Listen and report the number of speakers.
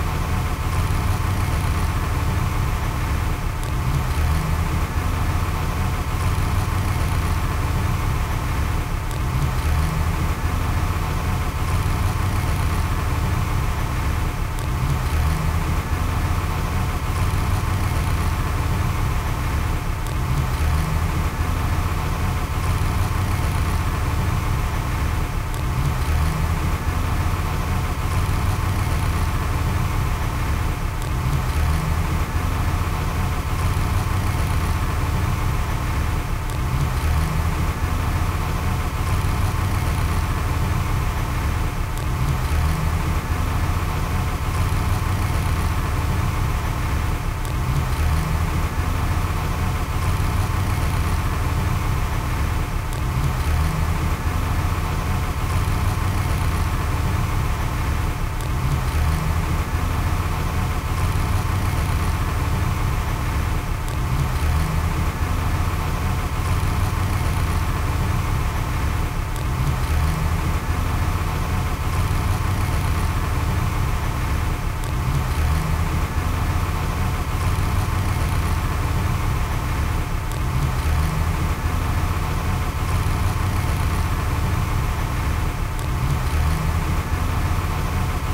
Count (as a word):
zero